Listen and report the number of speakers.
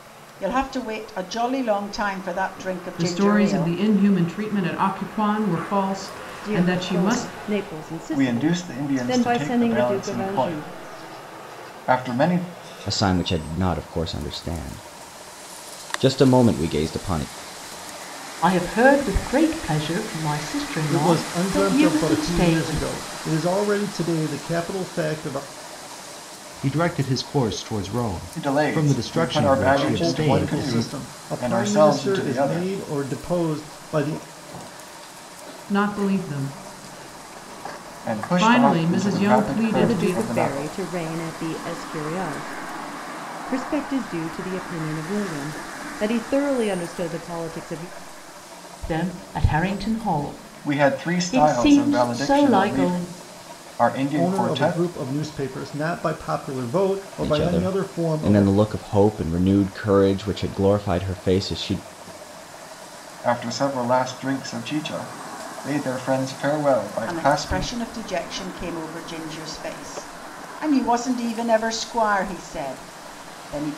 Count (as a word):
eight